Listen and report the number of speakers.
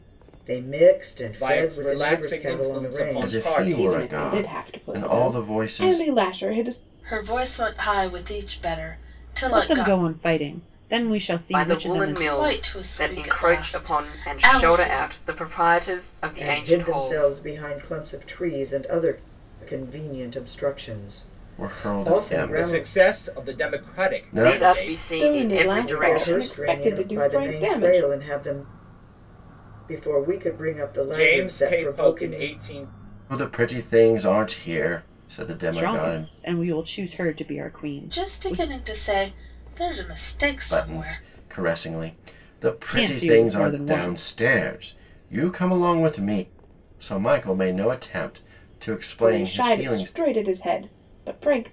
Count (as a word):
seven